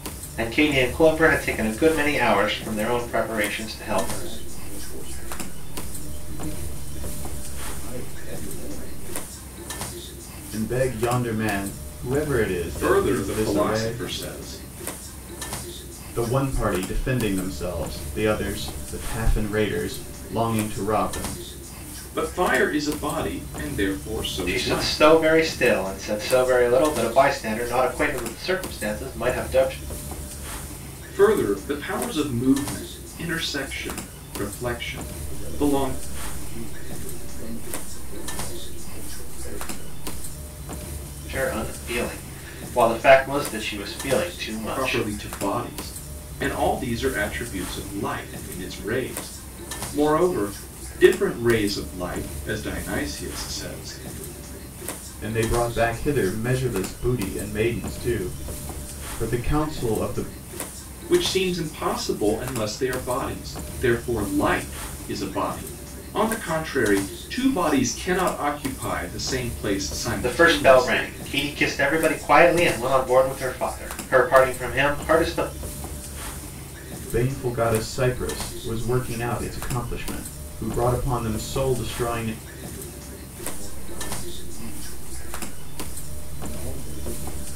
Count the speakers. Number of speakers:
4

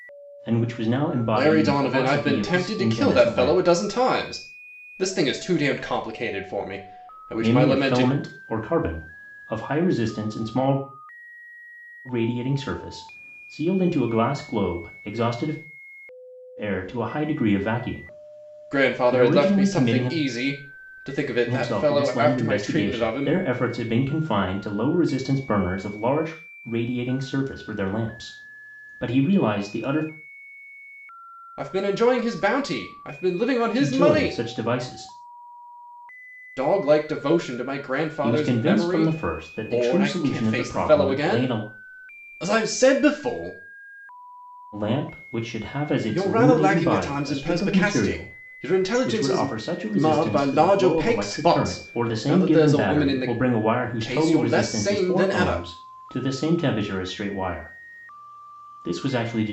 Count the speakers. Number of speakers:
2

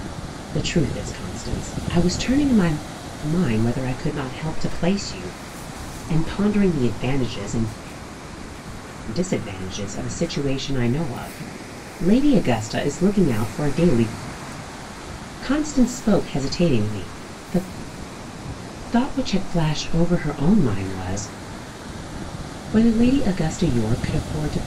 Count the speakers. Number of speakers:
1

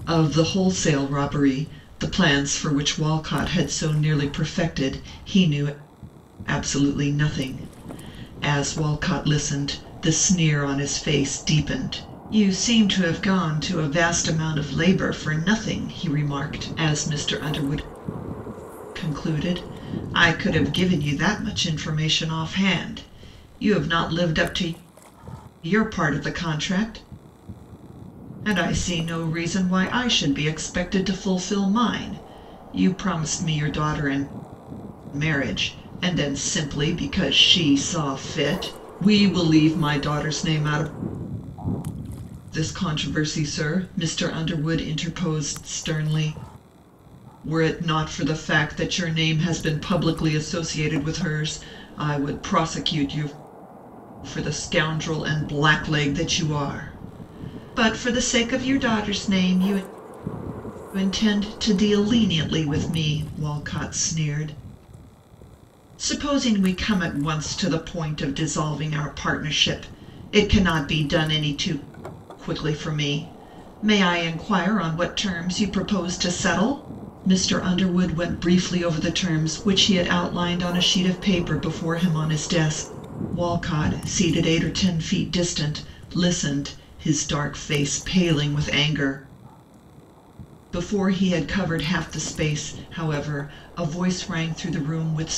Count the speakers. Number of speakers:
1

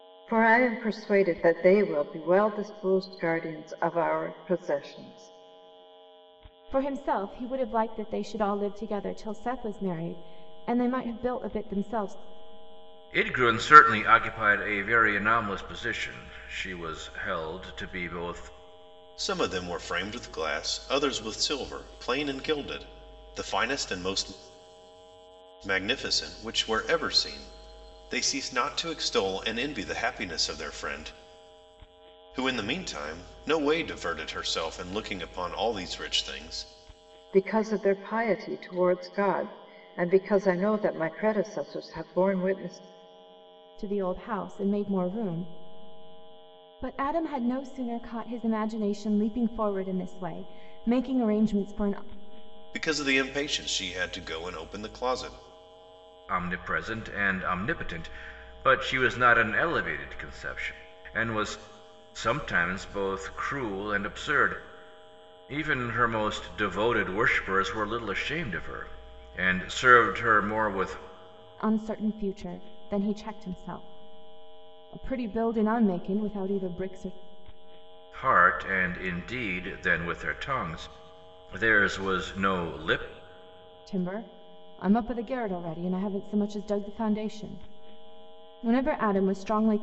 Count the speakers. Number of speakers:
4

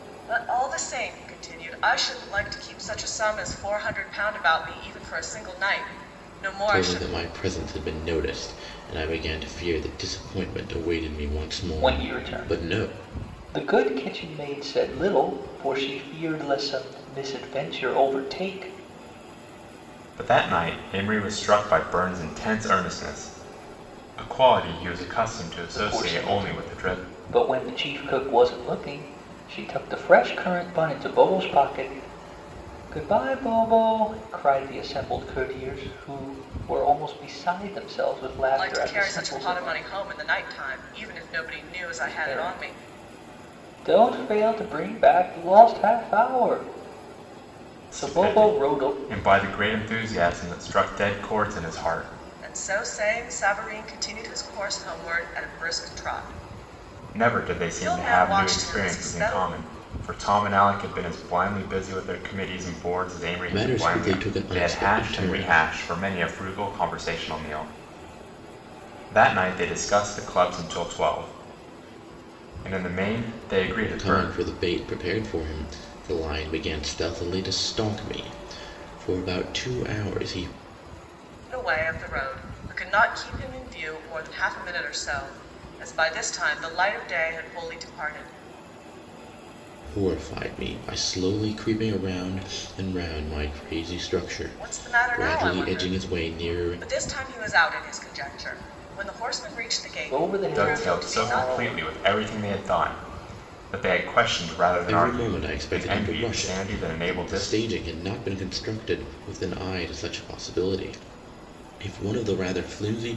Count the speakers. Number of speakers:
4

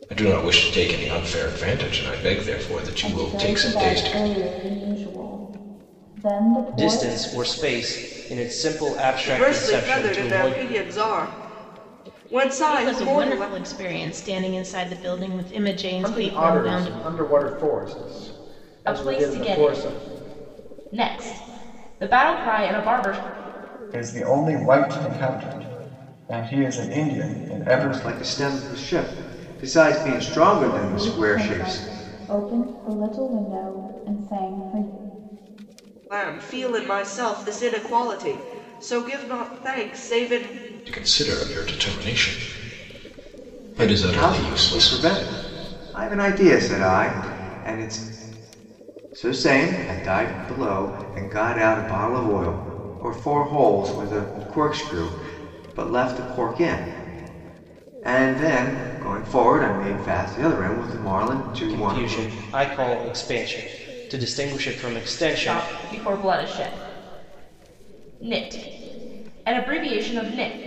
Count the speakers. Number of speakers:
9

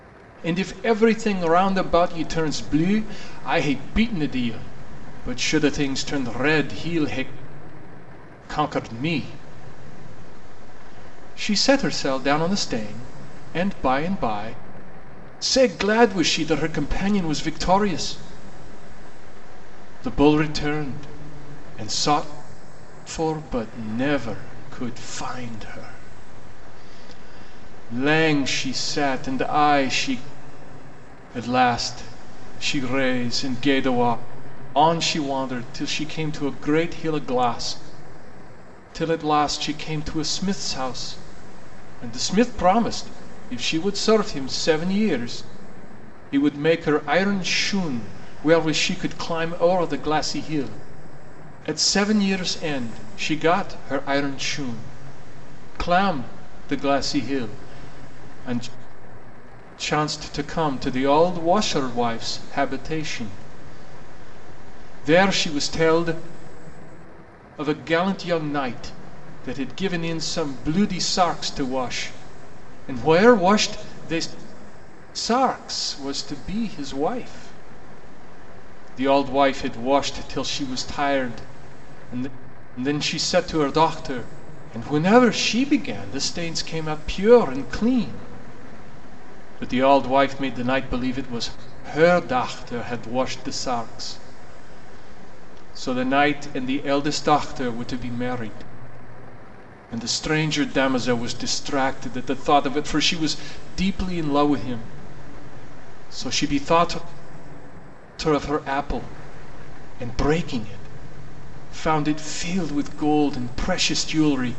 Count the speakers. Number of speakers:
1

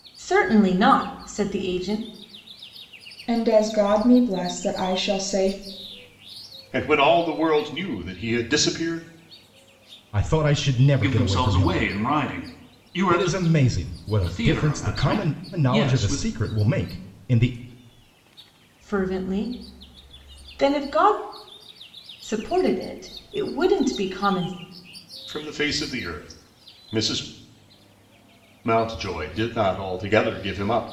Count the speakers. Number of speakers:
5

